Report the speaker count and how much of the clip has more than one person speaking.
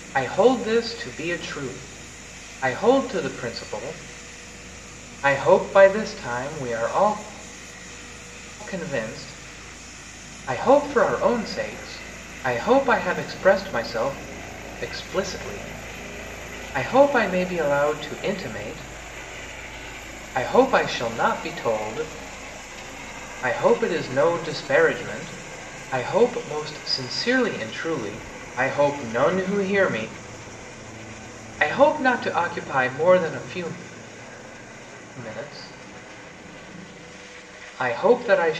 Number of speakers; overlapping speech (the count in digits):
1, no overlap